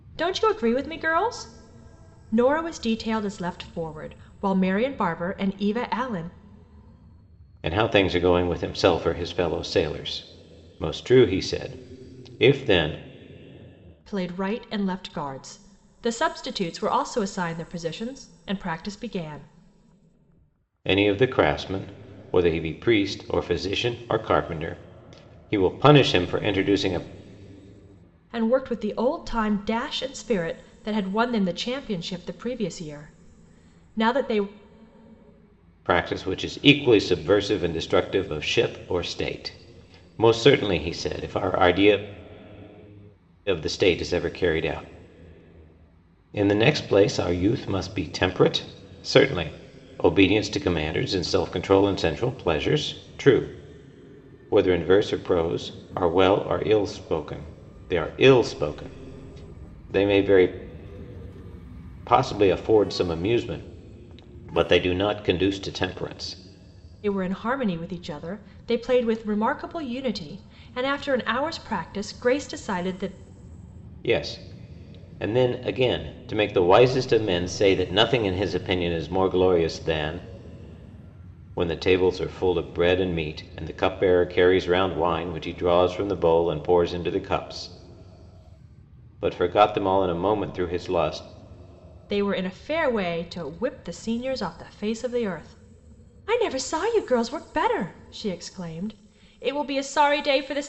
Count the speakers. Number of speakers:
2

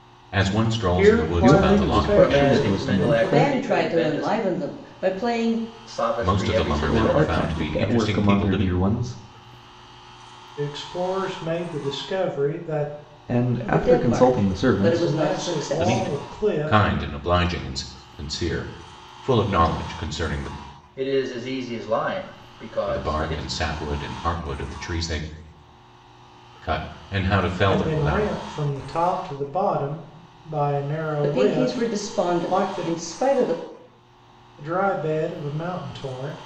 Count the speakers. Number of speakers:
5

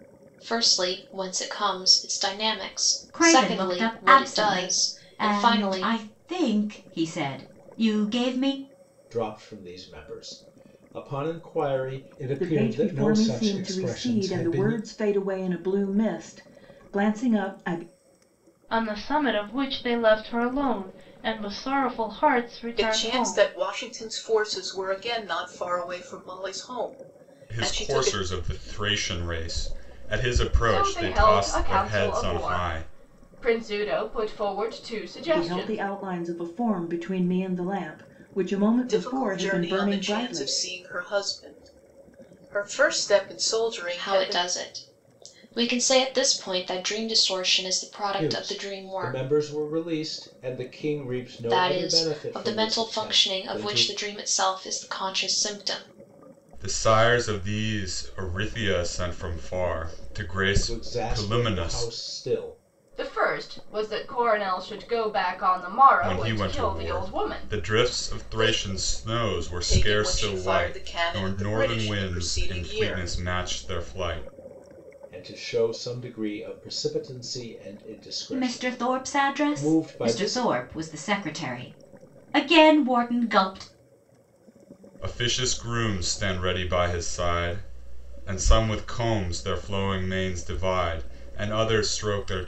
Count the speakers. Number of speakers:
8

